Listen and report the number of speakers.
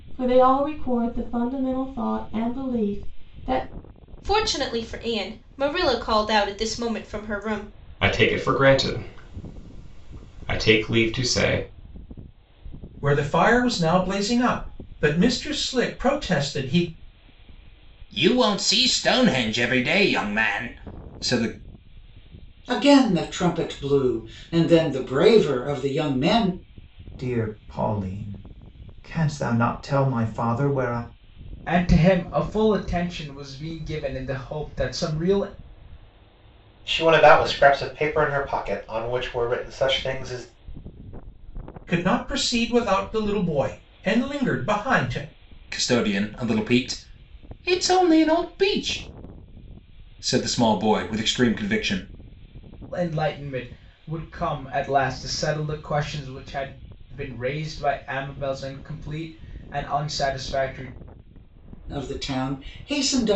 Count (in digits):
9